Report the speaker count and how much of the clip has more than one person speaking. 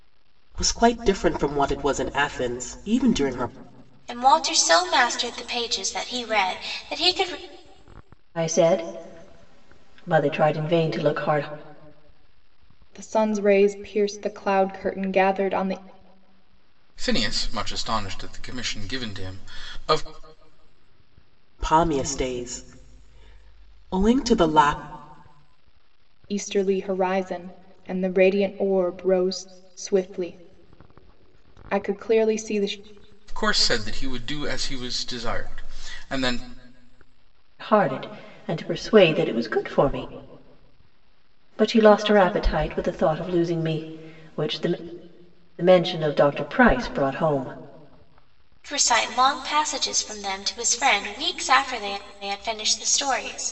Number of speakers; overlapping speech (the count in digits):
5, no overlap